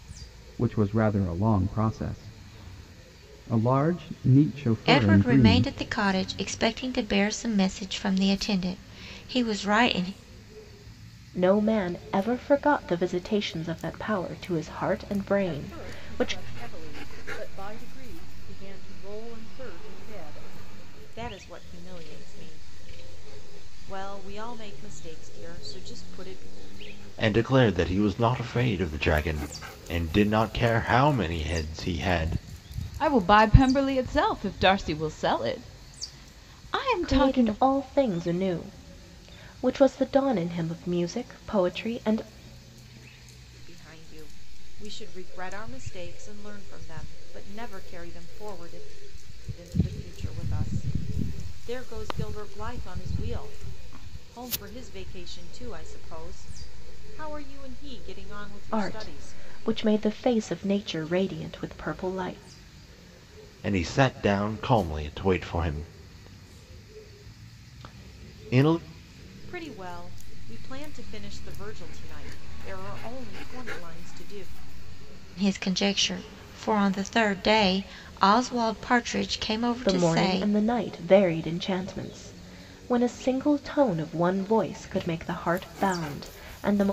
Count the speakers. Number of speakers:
7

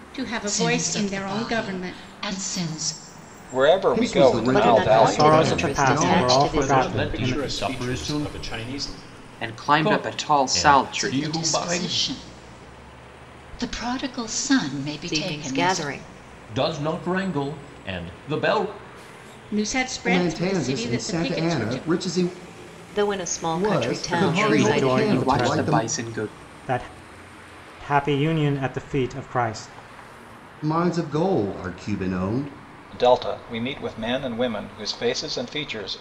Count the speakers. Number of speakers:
9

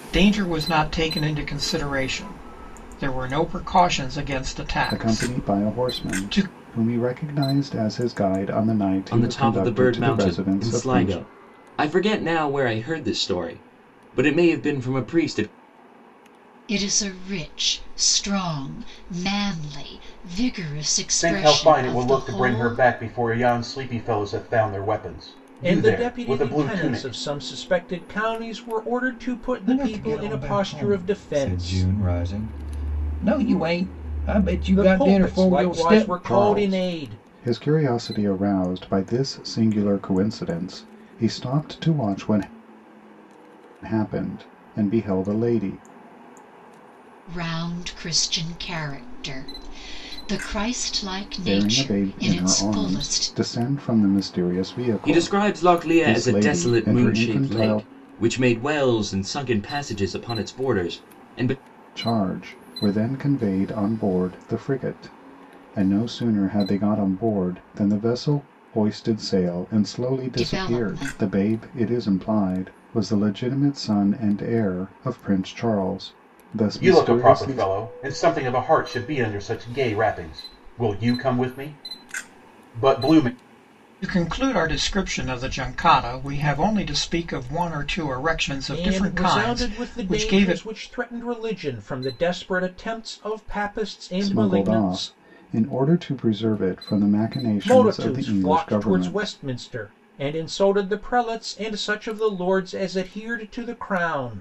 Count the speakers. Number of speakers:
7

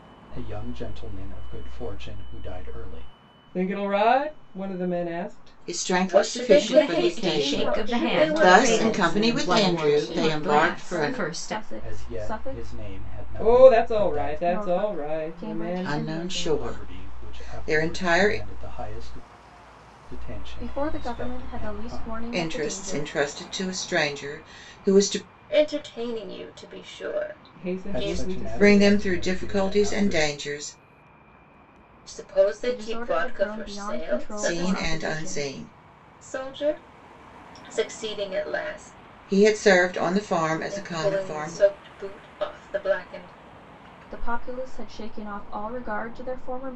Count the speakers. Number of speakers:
6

